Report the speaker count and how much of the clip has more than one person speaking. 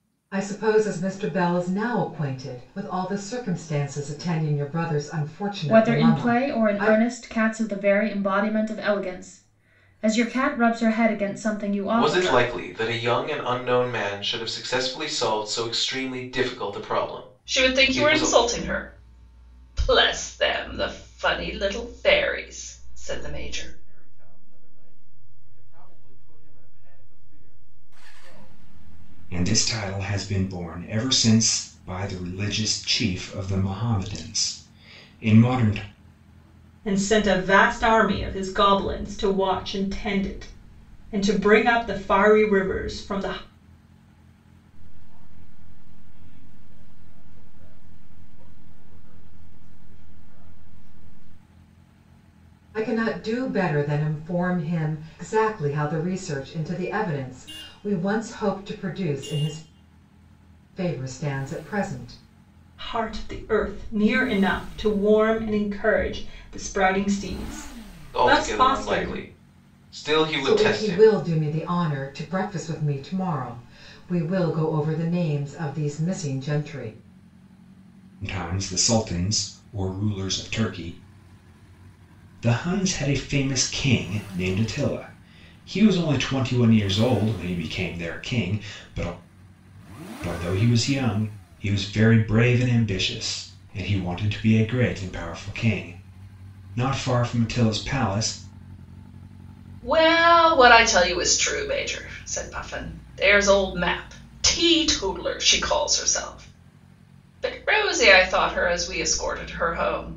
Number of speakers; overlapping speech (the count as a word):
seven, about 5%